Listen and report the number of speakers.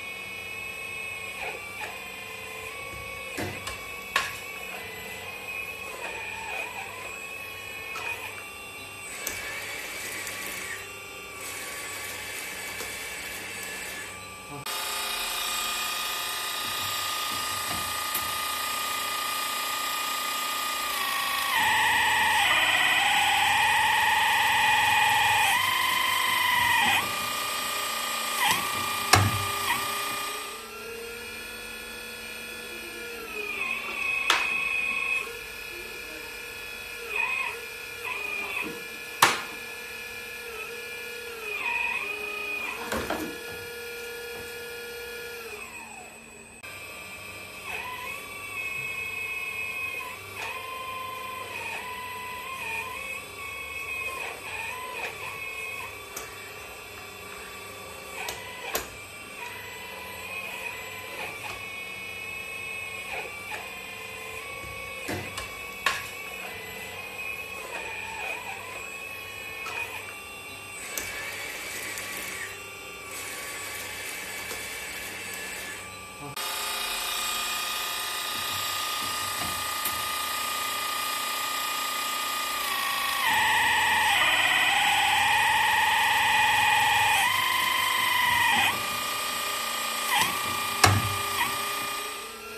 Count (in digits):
0